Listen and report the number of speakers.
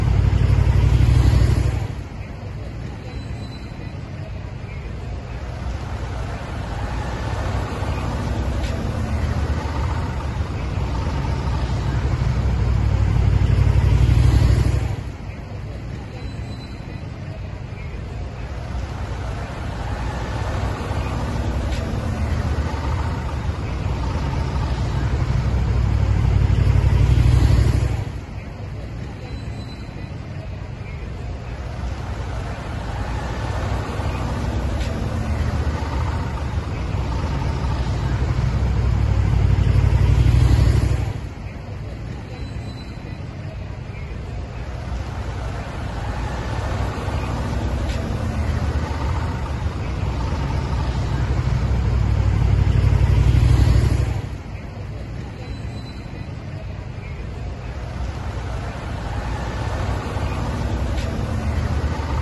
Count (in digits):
0